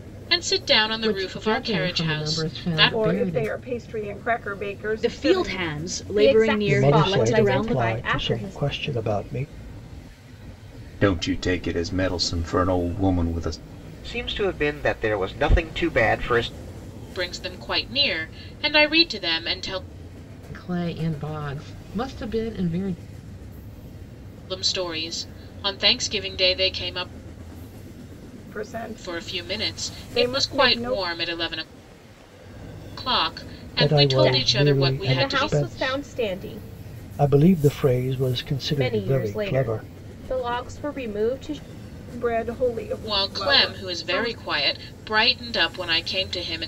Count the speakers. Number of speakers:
8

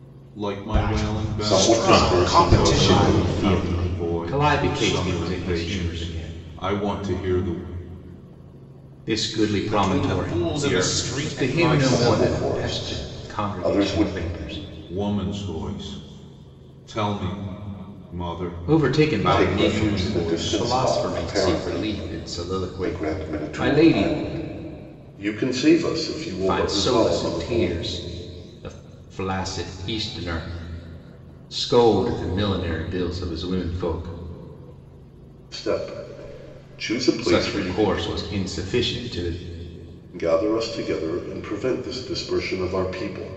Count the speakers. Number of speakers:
4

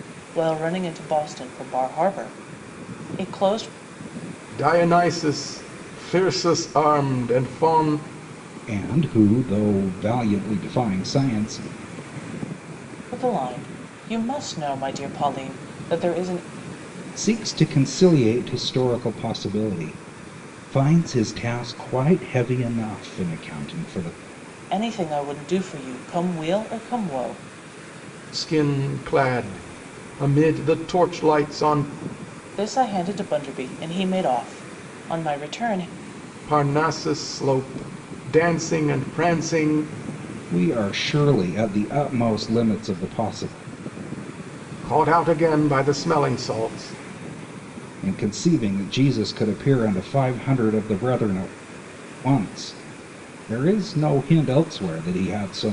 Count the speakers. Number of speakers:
3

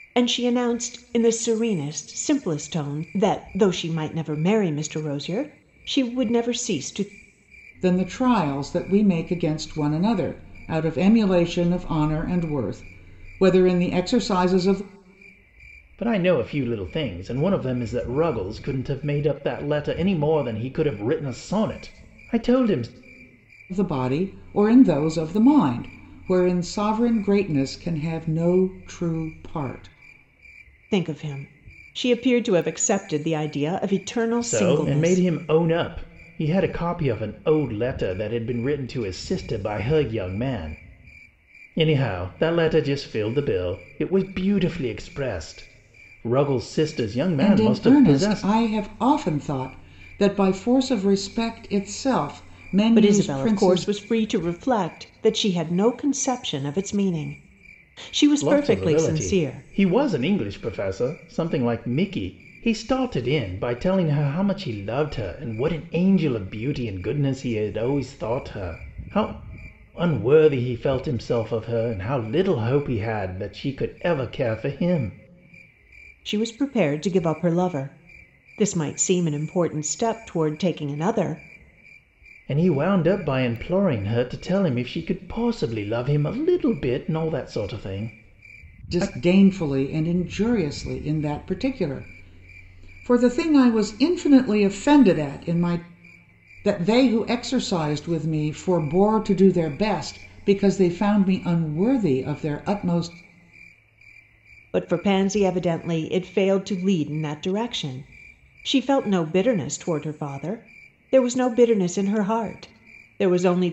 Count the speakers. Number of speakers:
3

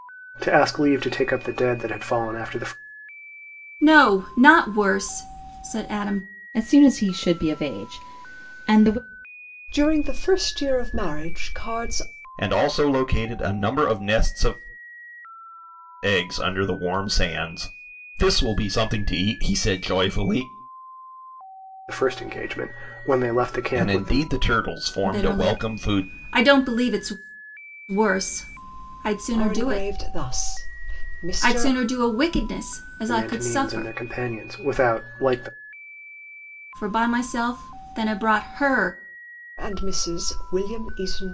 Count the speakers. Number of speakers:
5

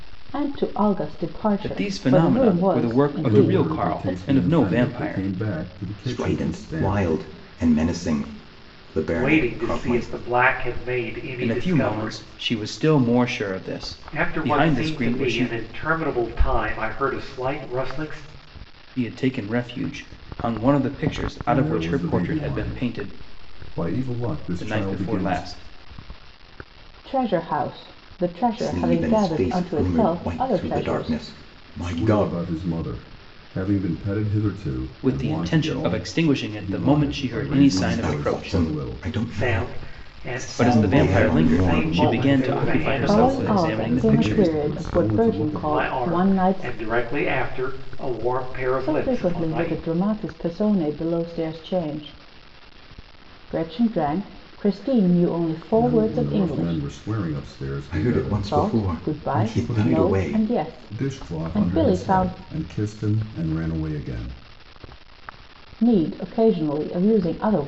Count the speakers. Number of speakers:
5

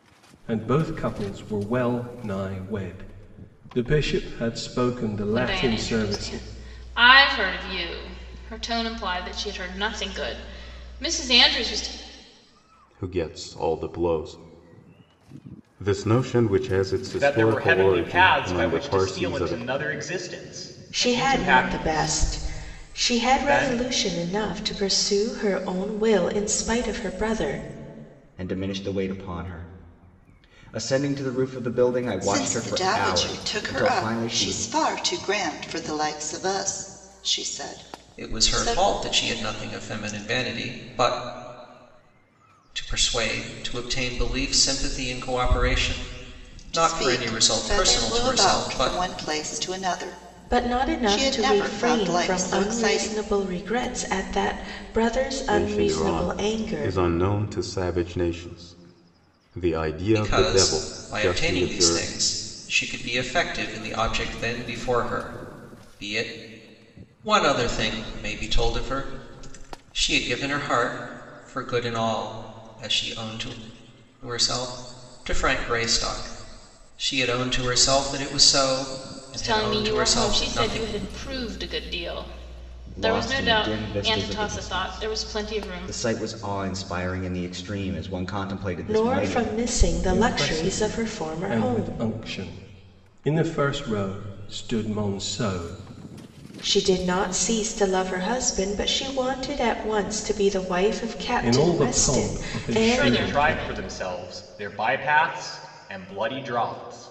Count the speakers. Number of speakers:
8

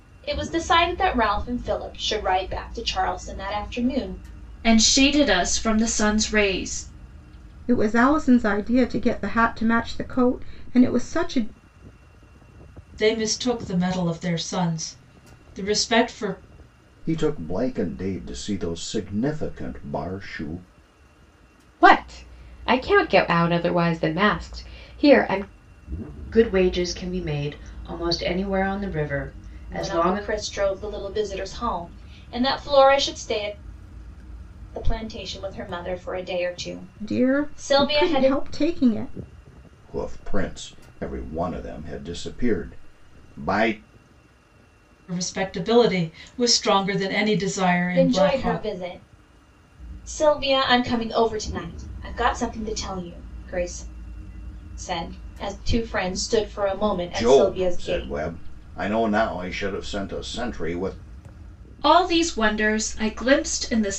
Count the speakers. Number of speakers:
7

